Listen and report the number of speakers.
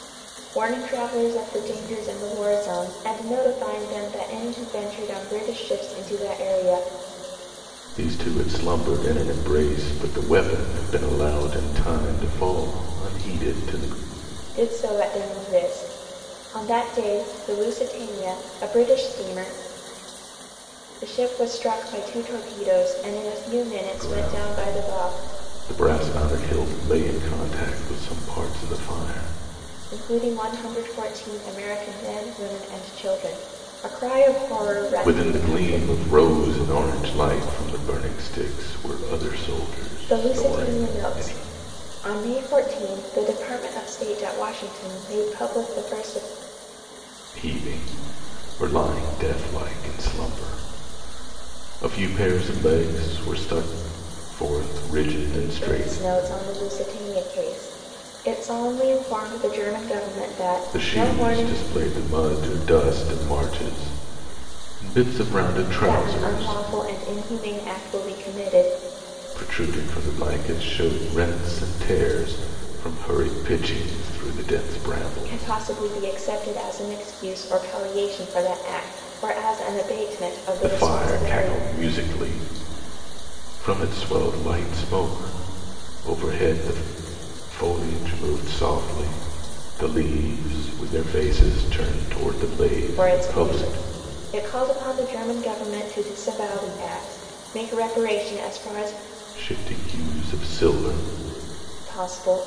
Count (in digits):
2